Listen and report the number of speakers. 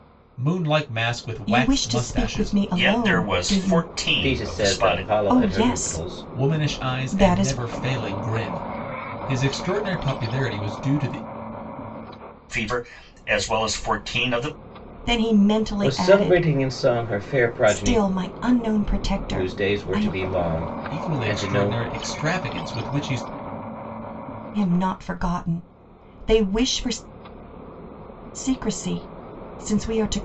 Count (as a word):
four